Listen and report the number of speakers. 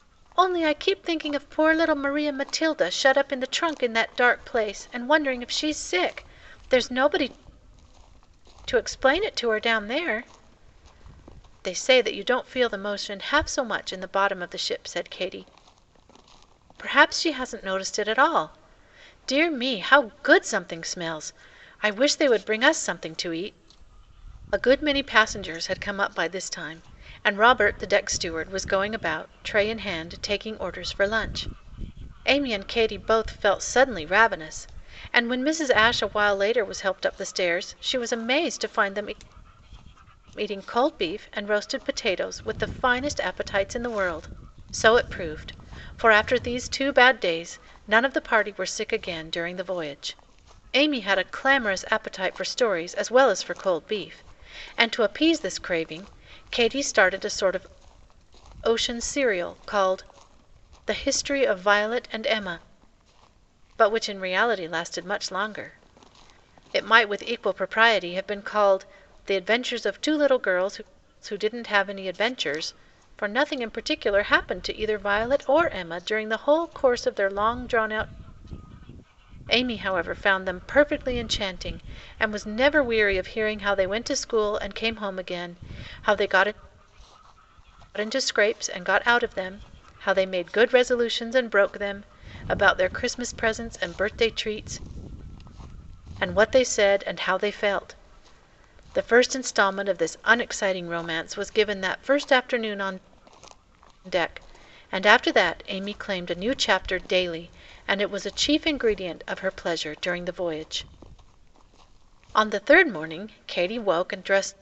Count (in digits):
1